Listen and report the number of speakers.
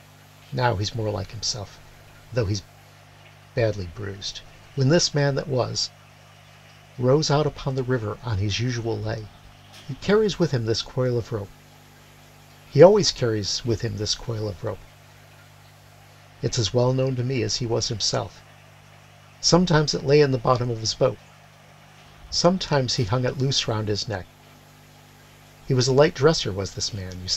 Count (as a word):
one